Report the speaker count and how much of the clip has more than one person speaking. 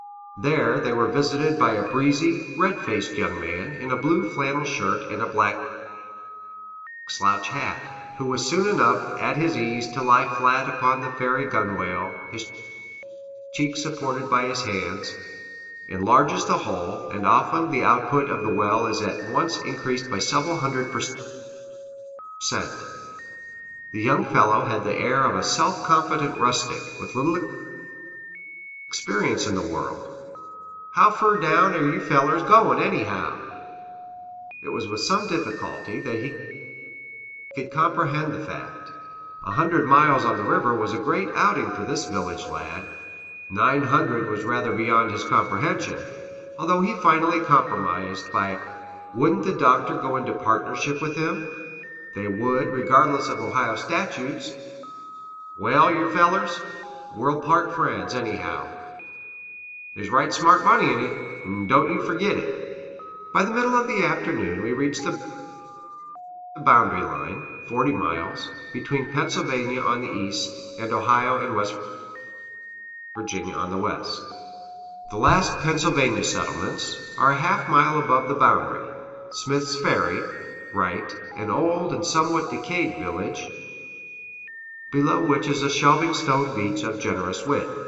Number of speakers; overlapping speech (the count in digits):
1, no overlap